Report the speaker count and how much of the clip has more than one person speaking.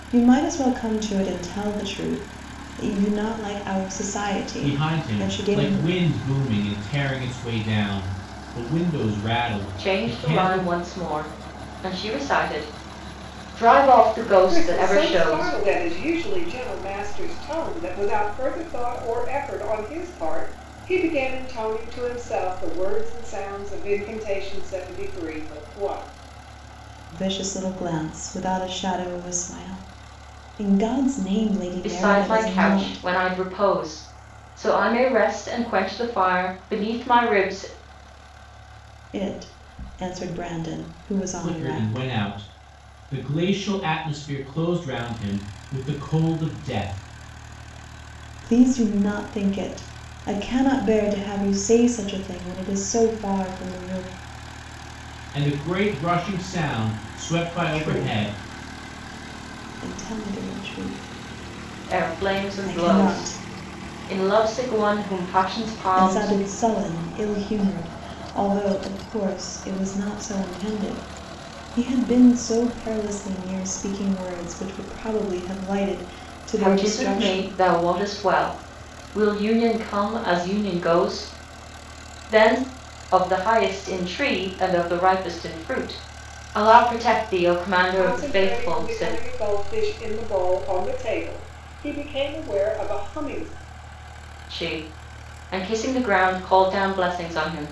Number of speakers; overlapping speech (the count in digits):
4, about 11%